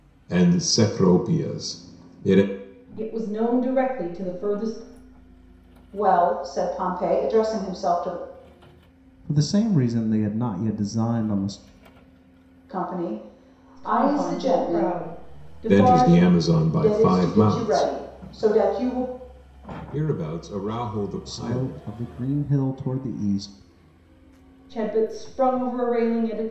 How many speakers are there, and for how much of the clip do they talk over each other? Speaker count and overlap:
four, about 13%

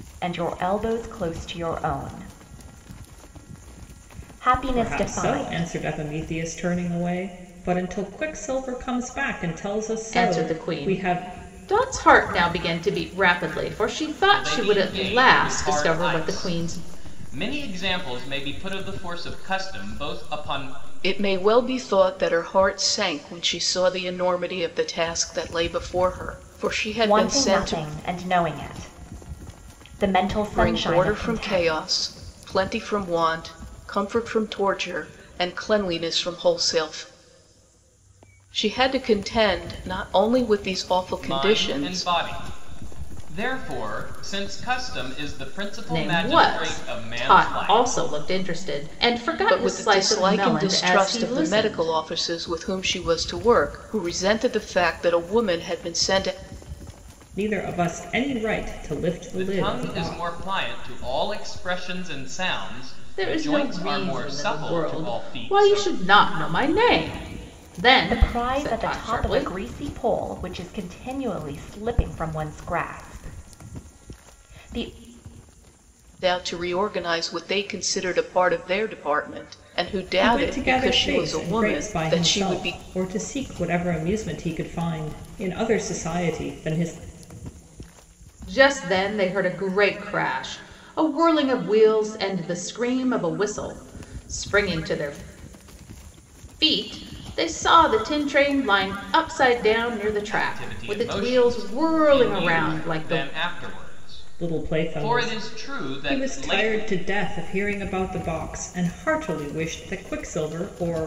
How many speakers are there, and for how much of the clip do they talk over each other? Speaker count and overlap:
five, about 23%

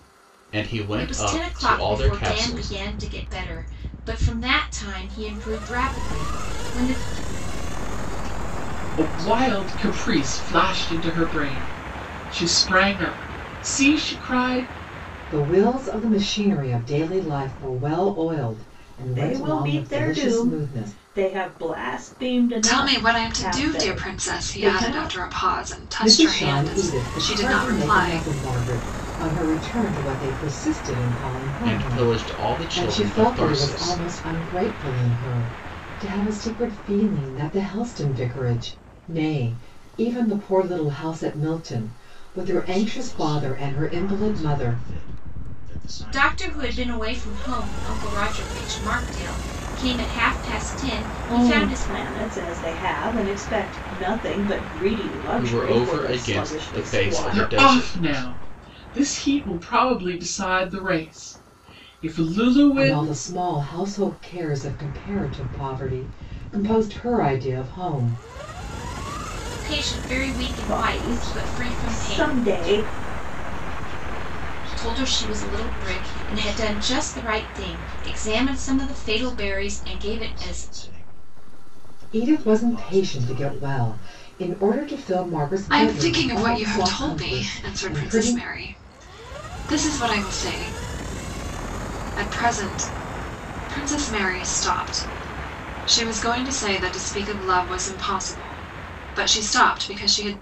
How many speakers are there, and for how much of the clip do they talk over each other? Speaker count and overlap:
seven, about 36%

